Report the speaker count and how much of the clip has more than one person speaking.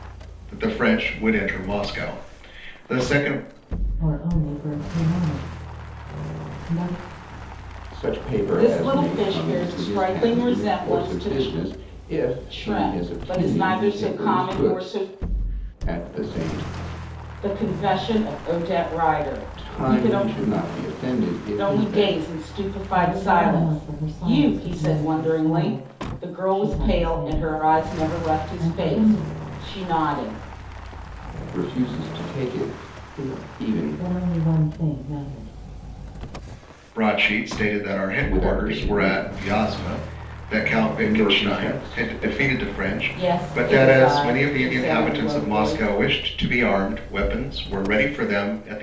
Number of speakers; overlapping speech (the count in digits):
4, about 39%